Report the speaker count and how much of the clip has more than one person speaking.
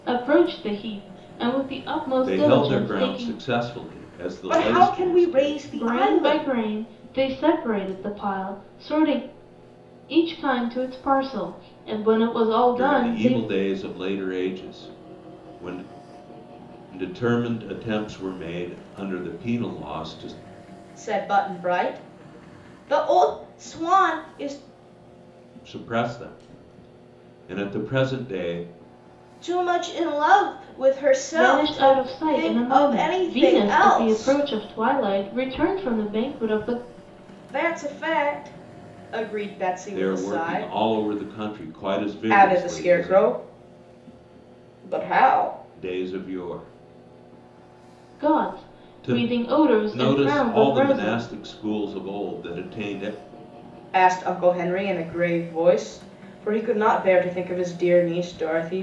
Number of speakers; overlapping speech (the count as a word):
three, about 20%